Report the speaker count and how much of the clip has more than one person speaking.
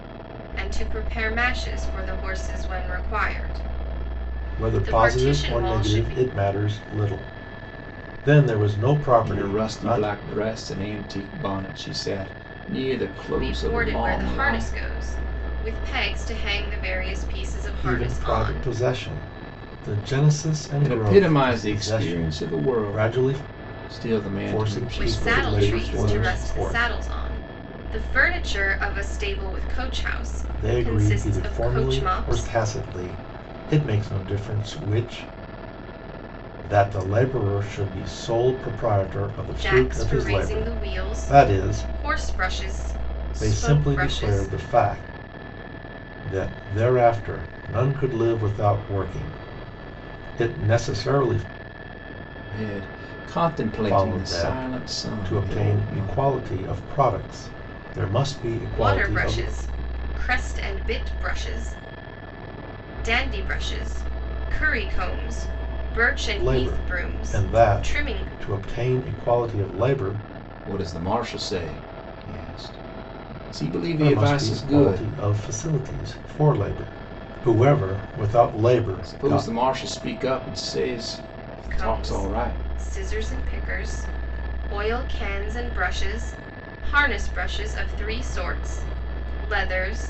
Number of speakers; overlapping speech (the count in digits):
3, about 28%